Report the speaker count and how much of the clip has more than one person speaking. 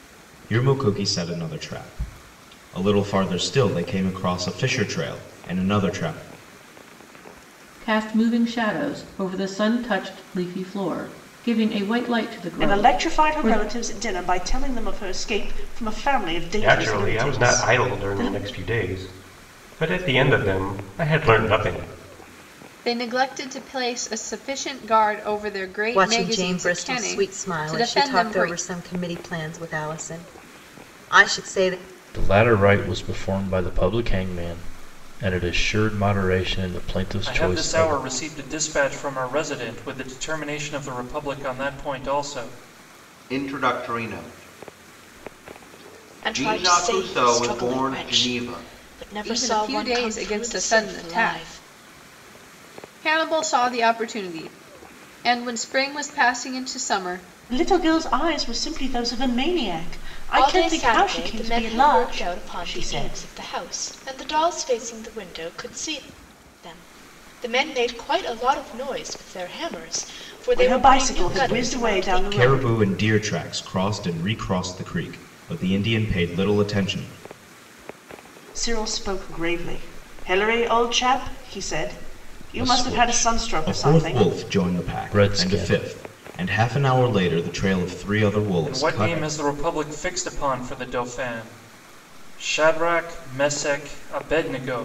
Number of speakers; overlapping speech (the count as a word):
ten, about 21%